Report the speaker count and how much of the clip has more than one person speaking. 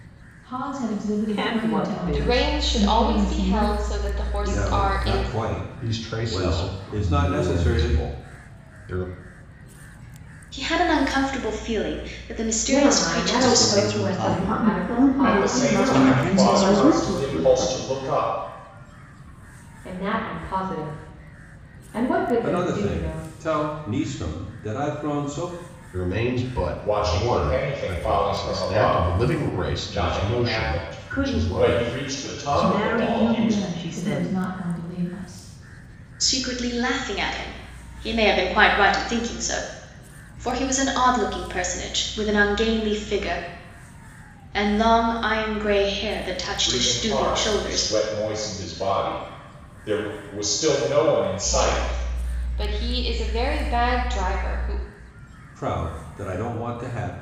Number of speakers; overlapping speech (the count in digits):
10, about 38%